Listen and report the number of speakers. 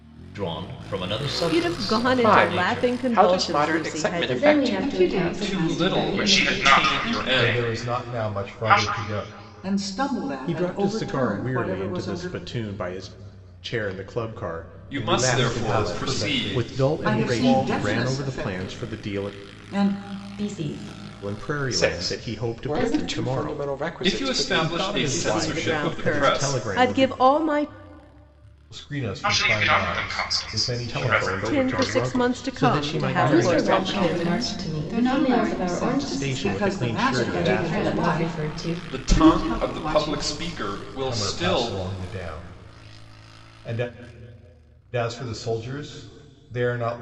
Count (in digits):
10